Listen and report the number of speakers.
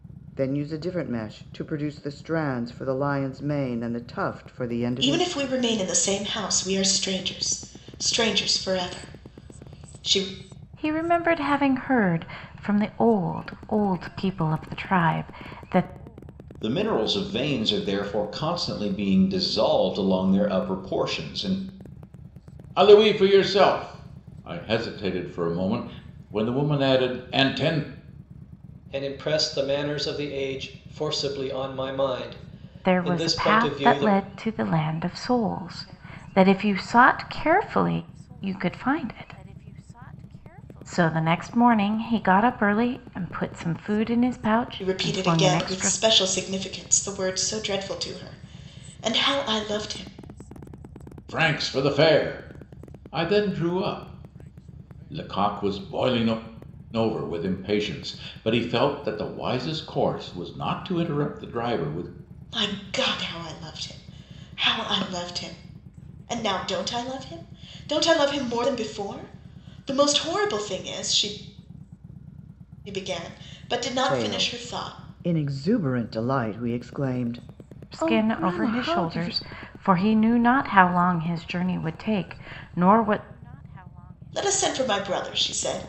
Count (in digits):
6